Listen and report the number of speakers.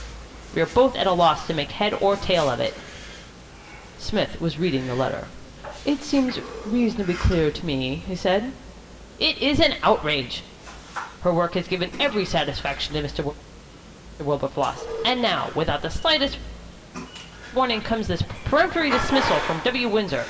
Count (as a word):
one